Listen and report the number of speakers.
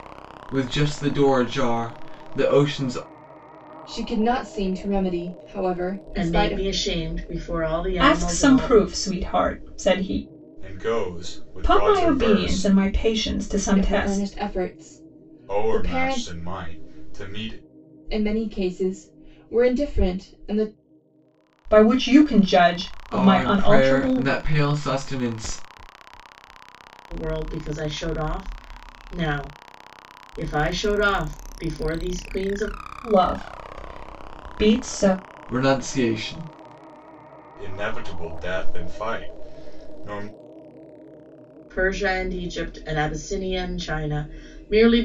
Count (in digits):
5